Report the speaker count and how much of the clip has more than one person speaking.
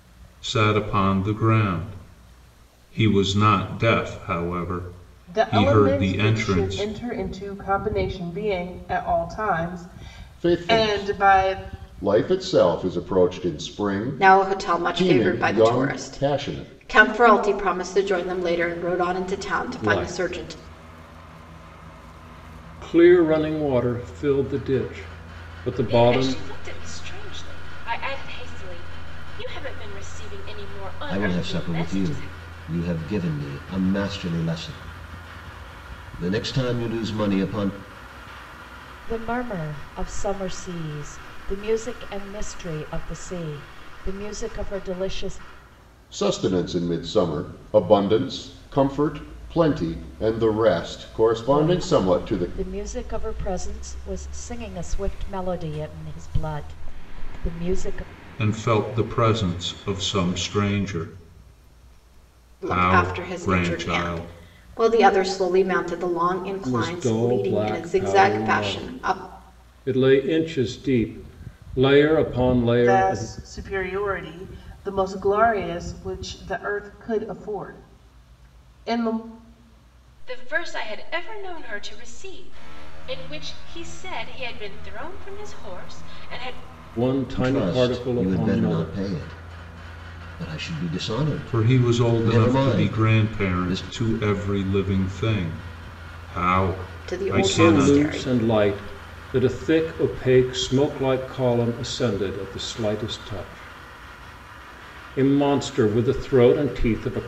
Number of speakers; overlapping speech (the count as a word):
eight, about 18%